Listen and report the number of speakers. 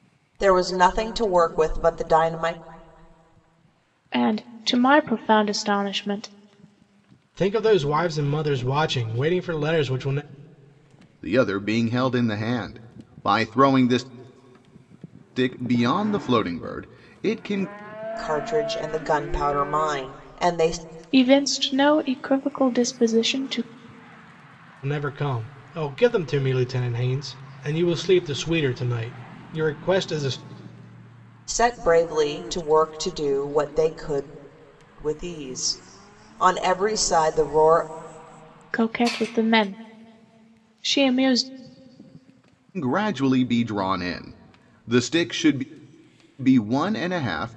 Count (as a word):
four